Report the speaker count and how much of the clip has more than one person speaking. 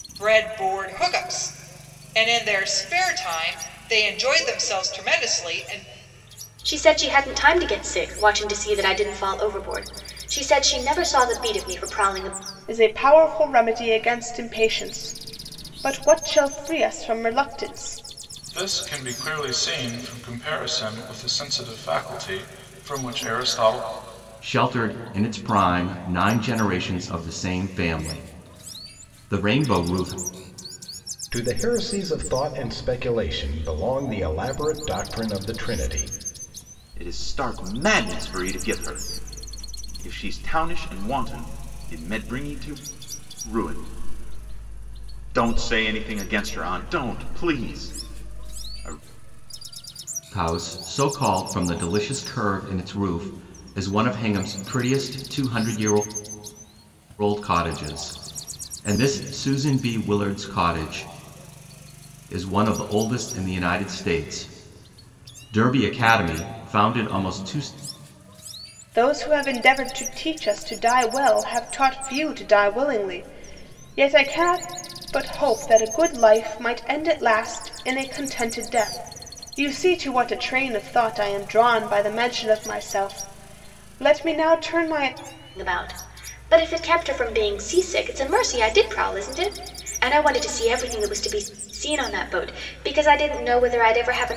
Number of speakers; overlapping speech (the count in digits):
7, no overlap